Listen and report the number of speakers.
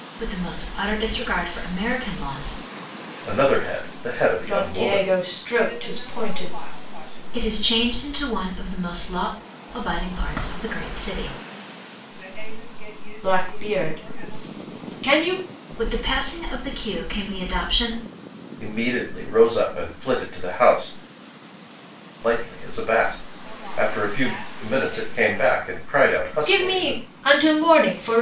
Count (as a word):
four